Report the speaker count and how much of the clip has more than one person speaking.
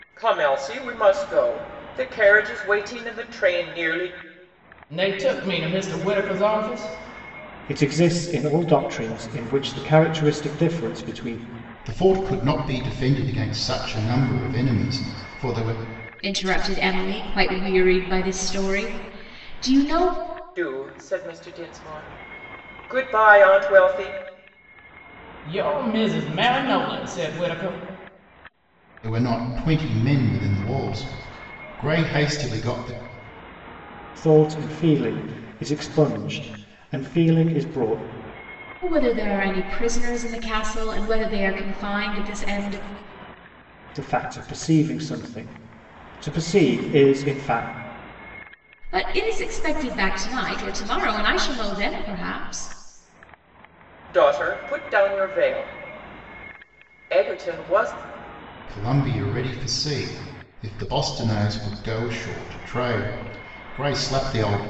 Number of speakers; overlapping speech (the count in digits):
5, no overlap